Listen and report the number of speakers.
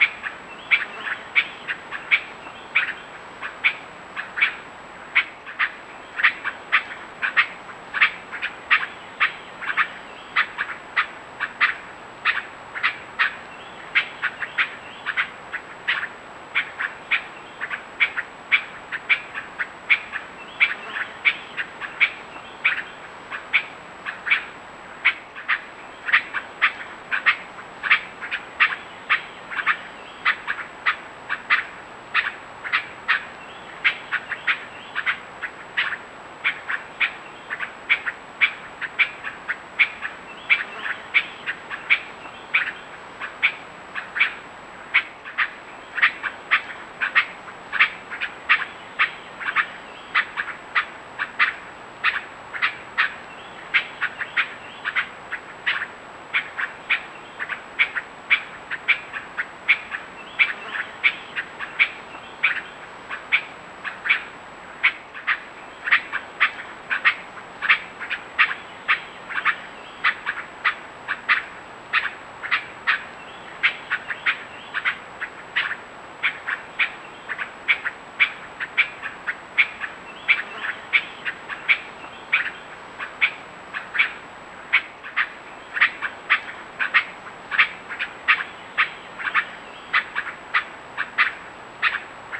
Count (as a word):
zero